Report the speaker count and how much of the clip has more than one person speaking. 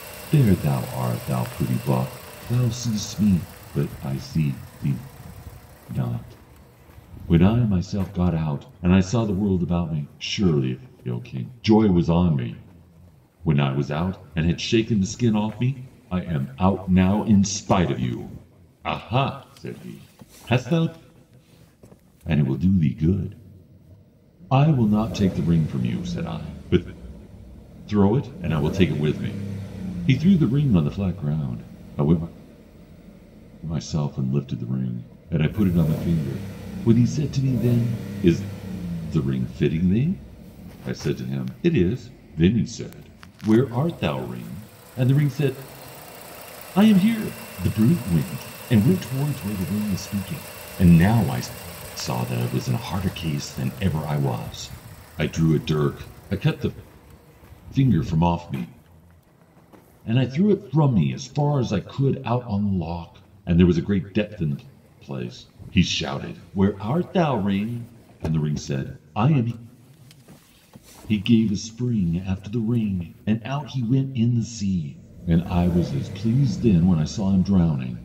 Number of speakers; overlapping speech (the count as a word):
one, no overlap